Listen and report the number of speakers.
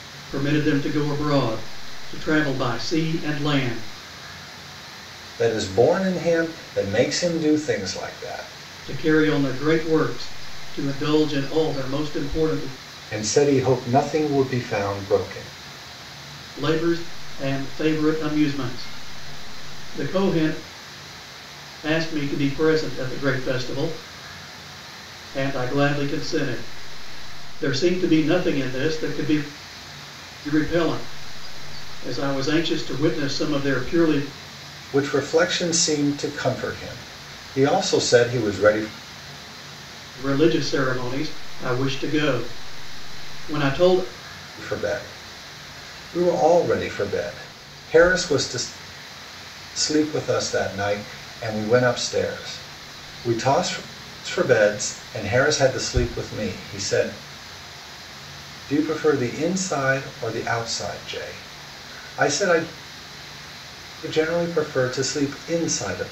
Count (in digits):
2